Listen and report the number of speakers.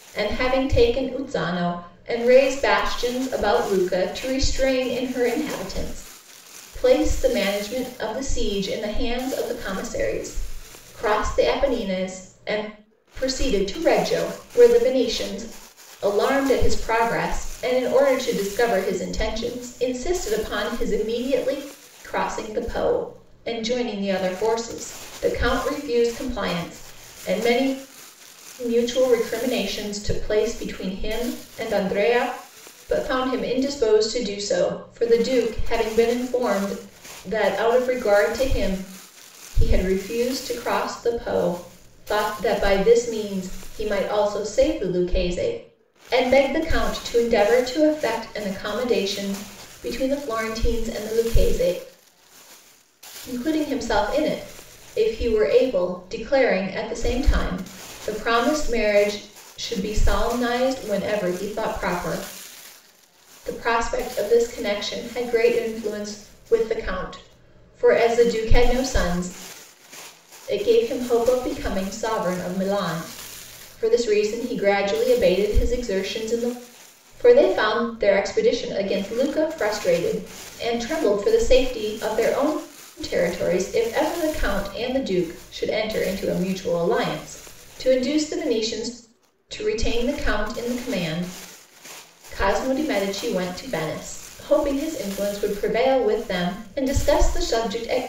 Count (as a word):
one